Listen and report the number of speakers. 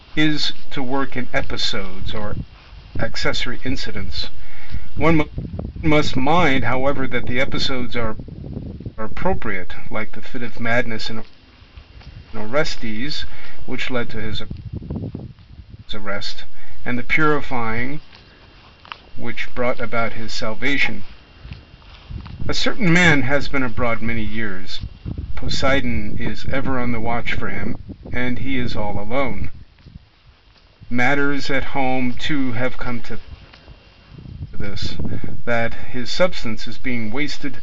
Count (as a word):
one